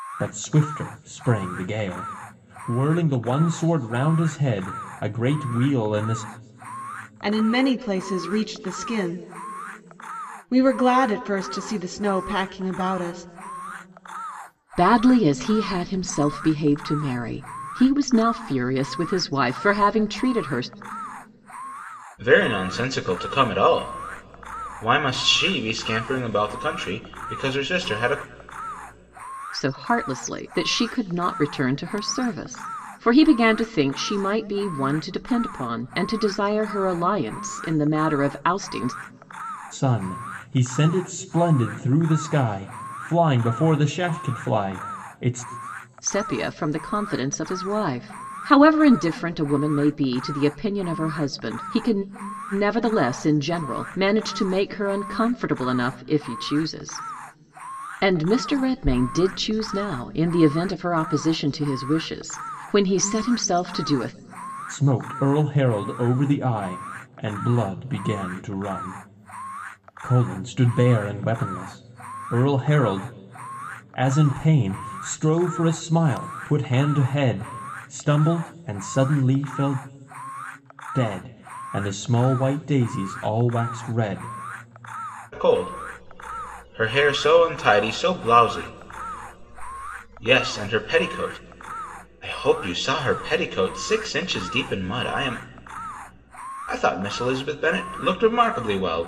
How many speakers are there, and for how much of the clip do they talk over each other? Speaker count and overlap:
4, no overlap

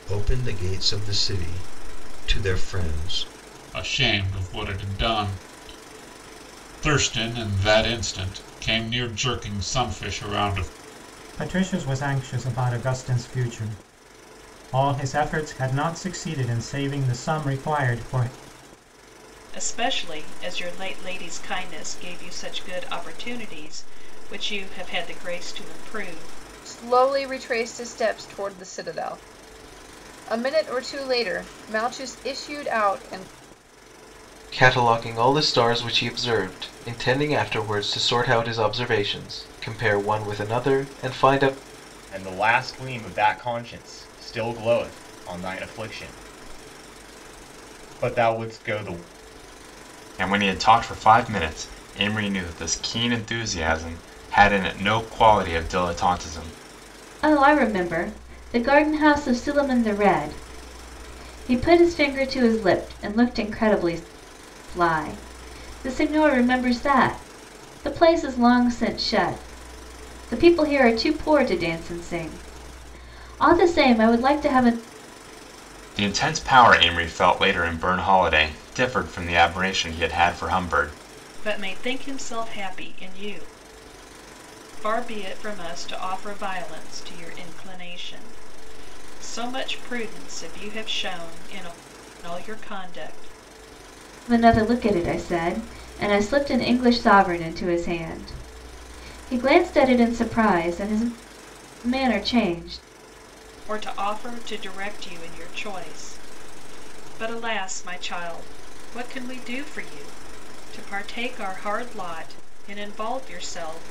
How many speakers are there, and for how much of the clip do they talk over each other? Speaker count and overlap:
9, no overlap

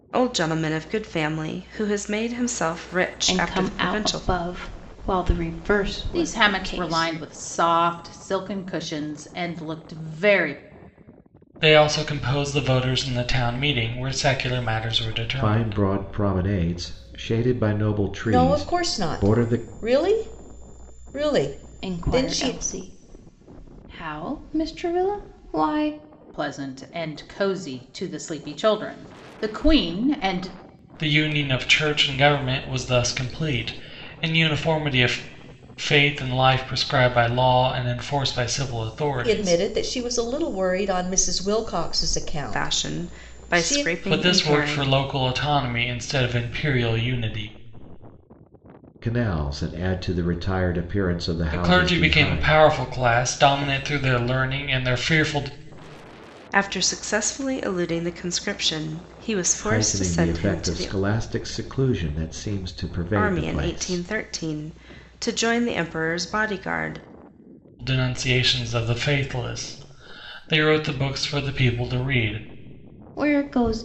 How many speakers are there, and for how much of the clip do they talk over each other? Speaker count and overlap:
6, about 15%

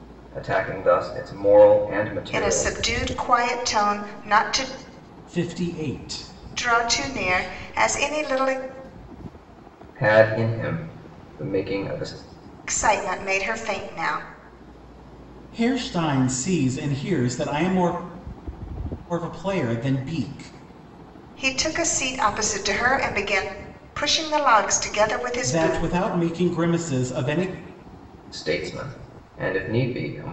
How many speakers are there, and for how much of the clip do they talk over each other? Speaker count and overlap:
3, about 7%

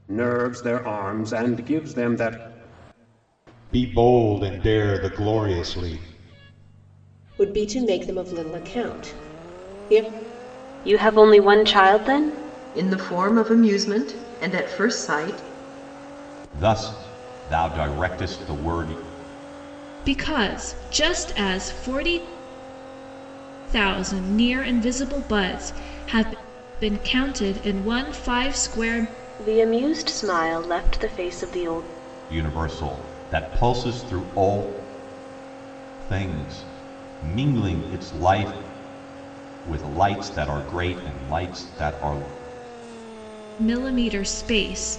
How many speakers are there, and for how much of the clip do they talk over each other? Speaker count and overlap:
7, no overlap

